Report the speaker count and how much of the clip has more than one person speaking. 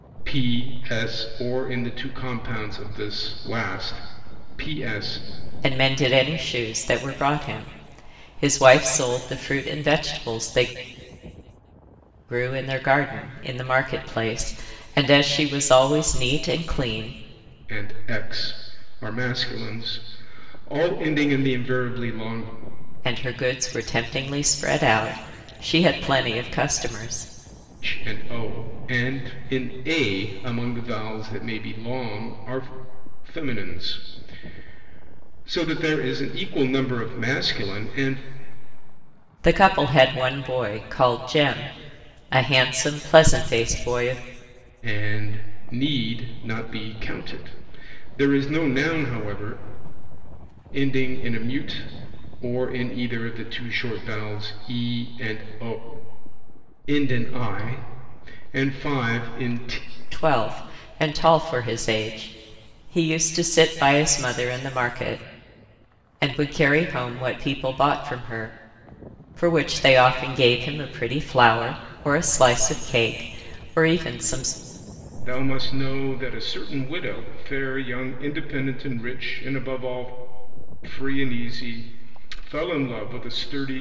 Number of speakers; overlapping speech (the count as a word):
two, no overlap